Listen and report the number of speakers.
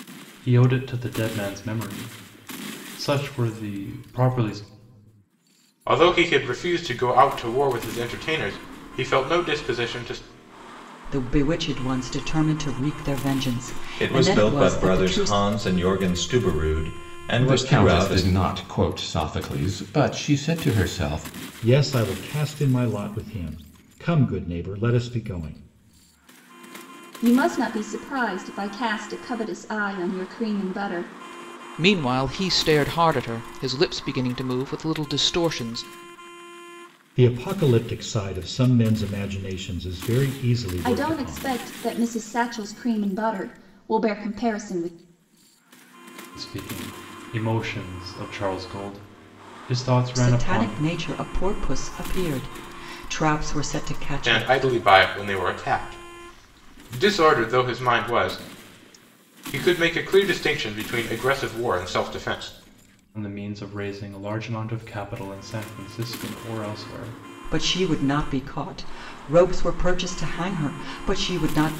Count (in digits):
8